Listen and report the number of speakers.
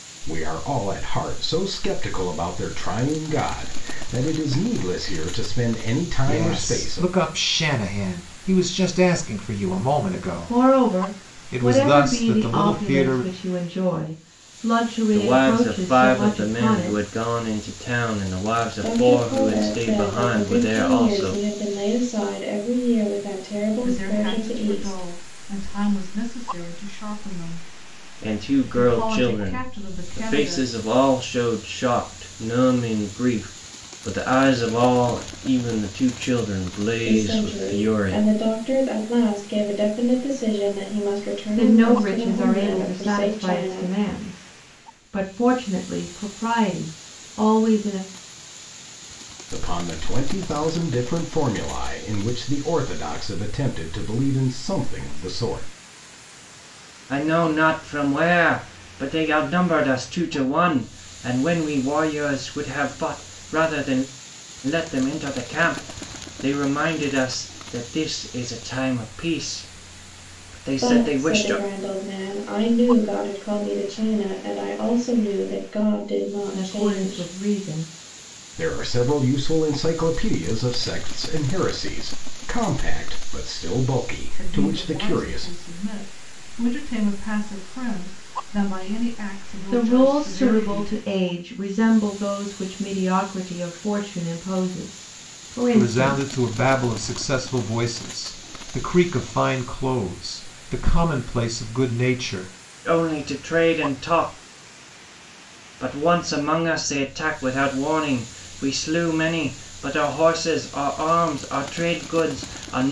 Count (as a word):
six